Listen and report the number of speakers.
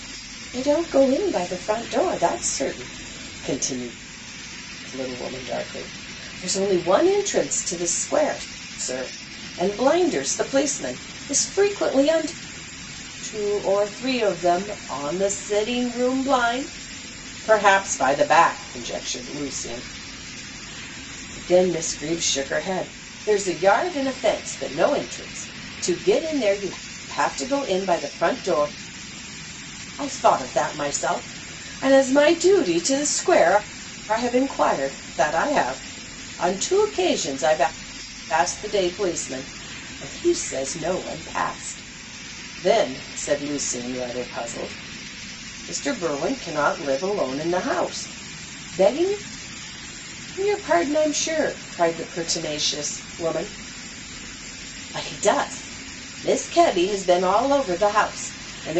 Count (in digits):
1